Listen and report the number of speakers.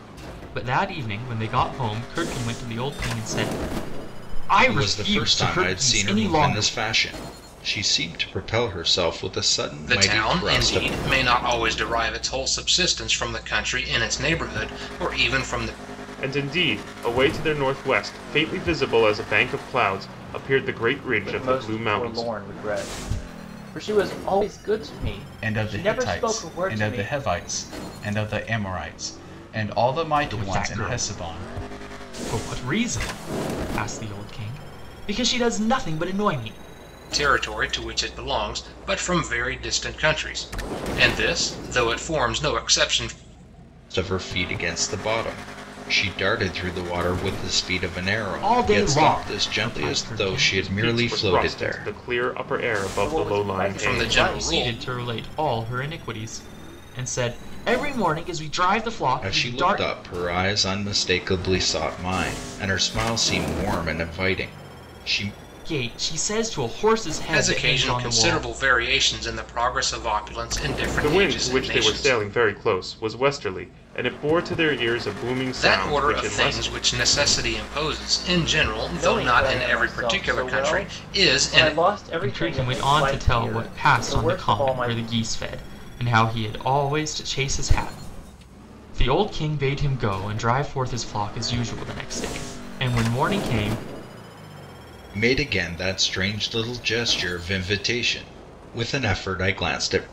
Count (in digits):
6